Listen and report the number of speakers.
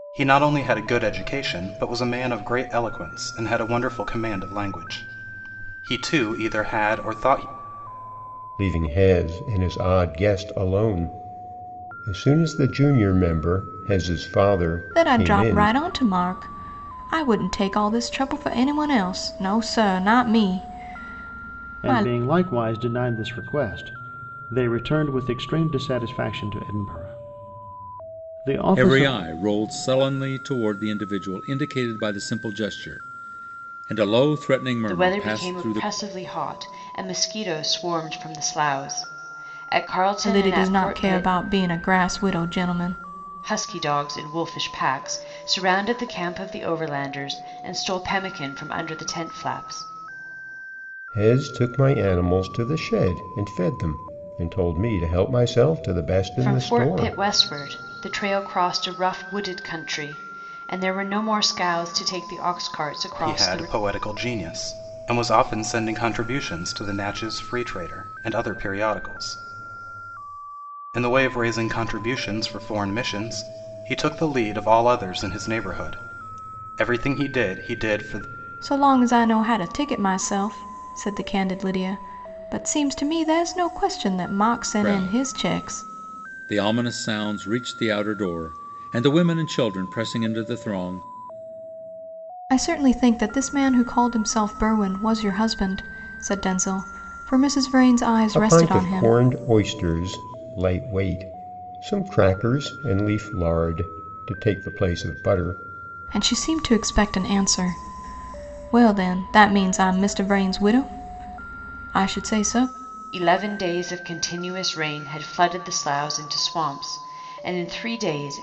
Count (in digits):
6